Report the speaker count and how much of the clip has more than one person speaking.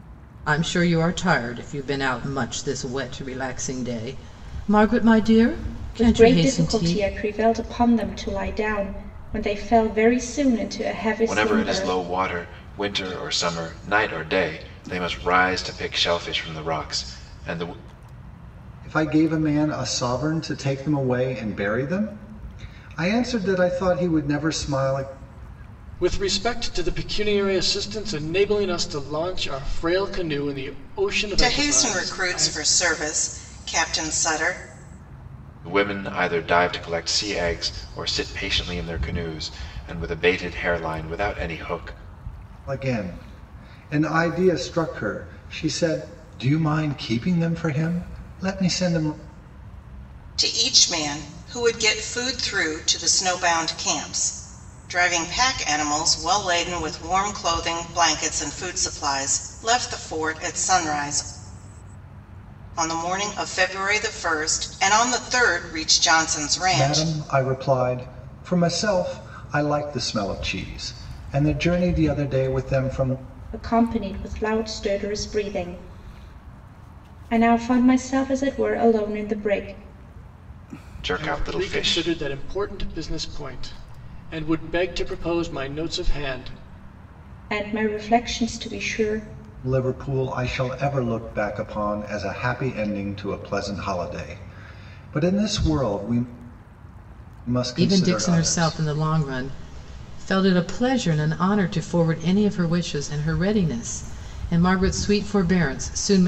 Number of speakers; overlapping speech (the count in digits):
6, about 5%